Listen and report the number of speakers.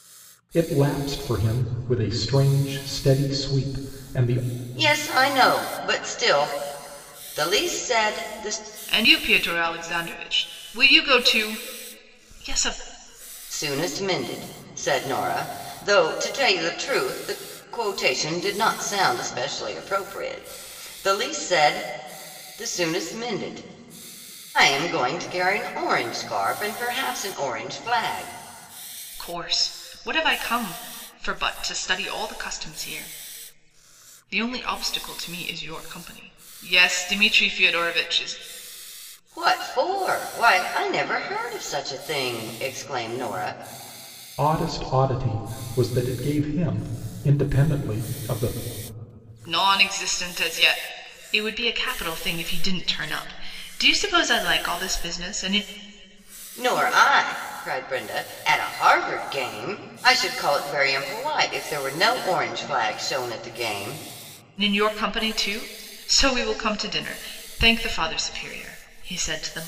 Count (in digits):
3